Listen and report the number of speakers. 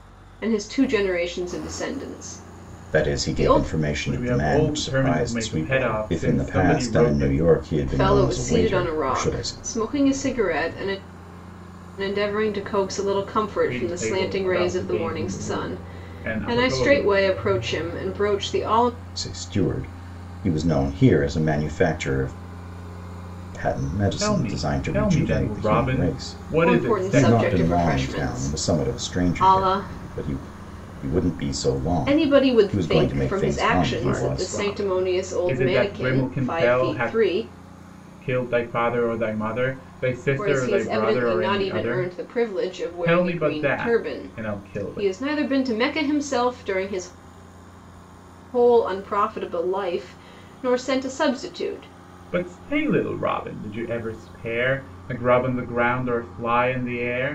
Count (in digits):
3